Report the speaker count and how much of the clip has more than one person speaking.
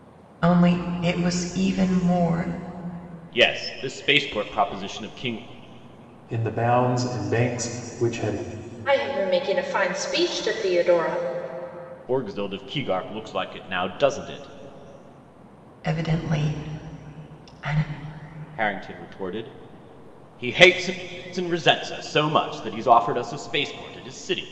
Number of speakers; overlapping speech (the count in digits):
4, no overlap